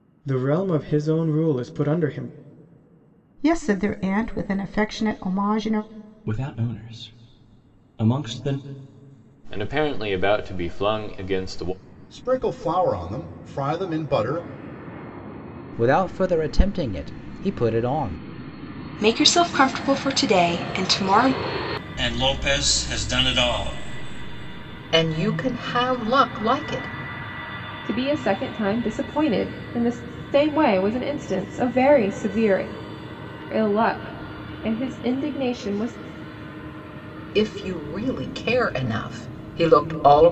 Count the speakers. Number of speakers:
ten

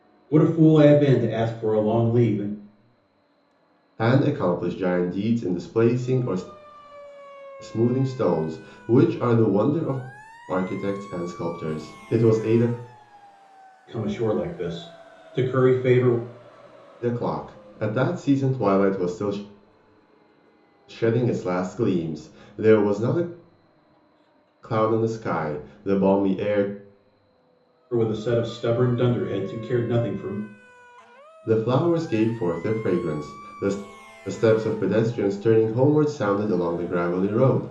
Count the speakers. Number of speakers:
two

